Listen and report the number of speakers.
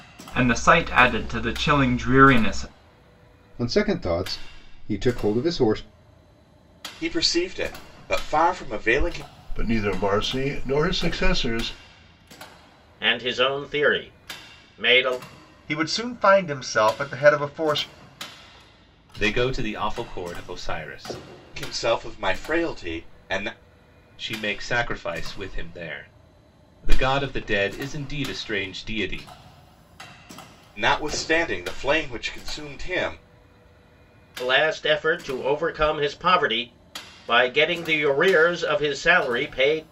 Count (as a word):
seven